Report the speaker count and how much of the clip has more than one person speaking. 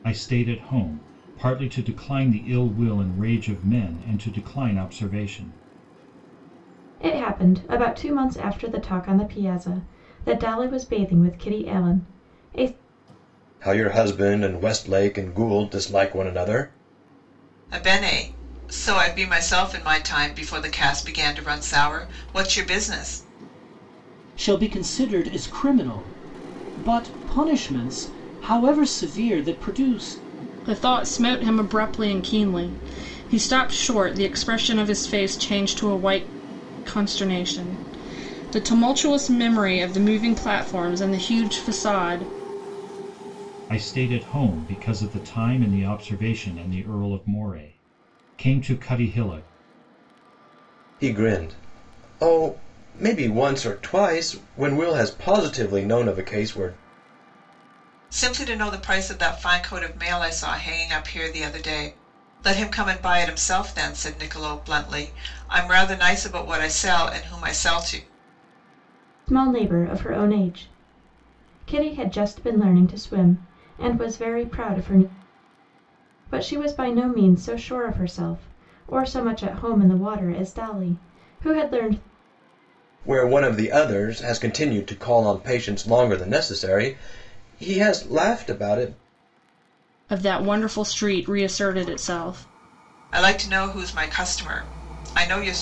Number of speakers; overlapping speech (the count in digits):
6, no overlap